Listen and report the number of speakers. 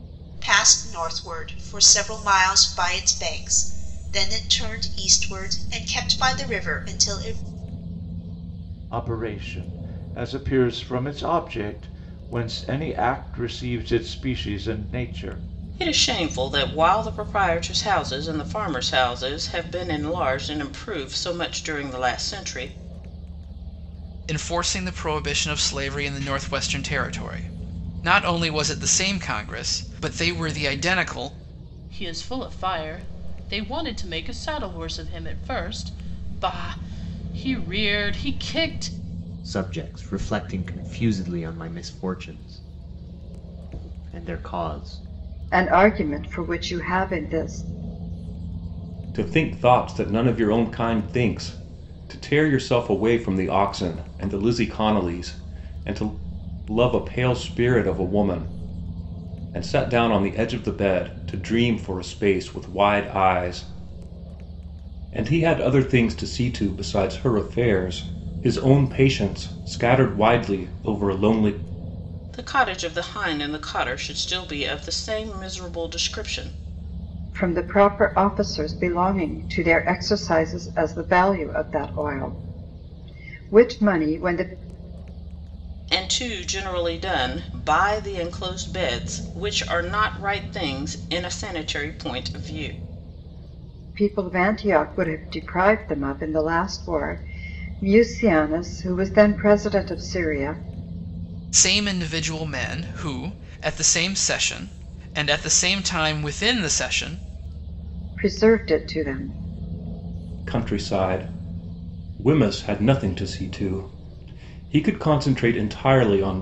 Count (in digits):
8